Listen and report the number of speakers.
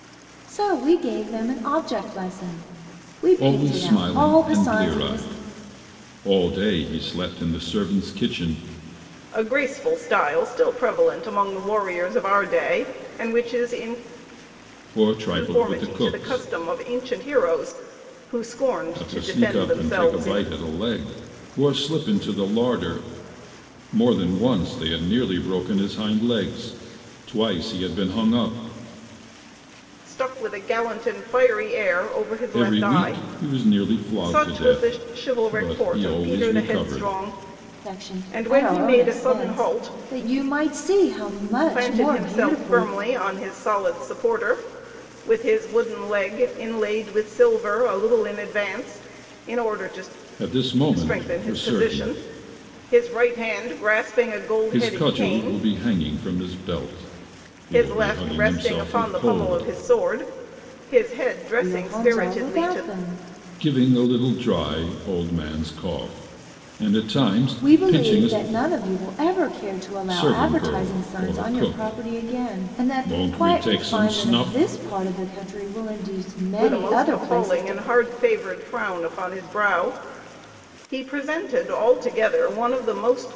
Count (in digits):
3